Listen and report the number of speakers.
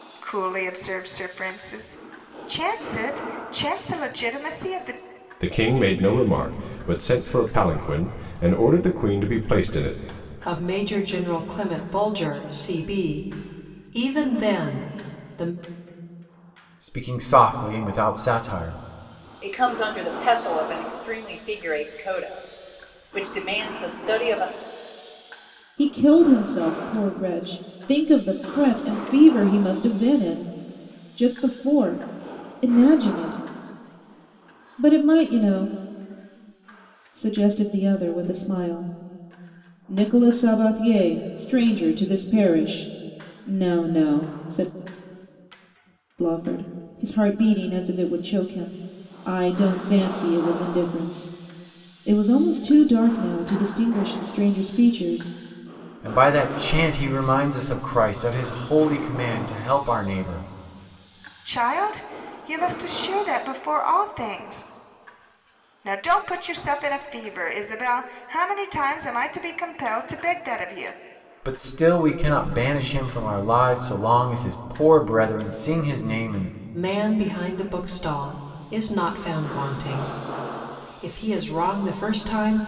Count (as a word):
six